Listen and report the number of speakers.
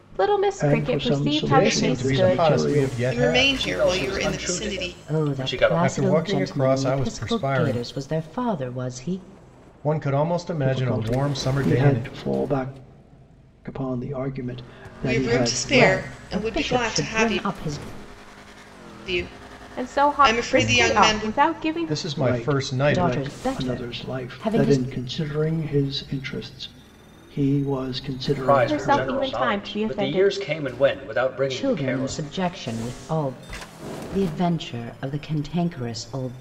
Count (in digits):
6